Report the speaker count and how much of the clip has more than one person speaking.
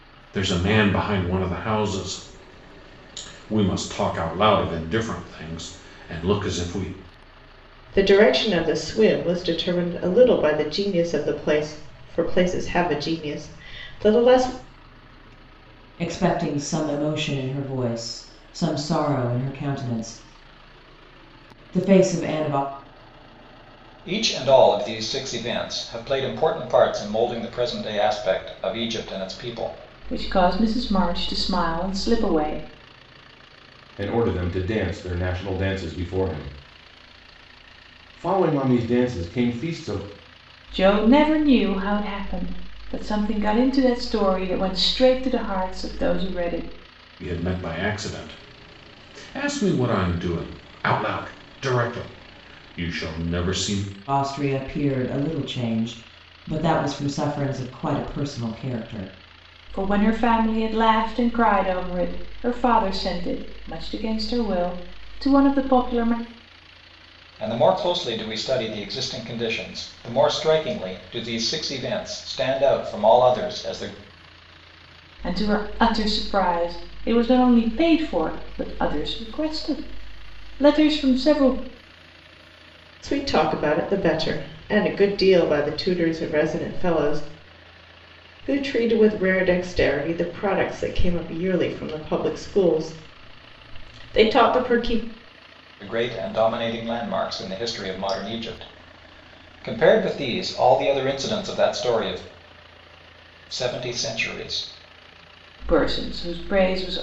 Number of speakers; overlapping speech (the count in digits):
6, no overlap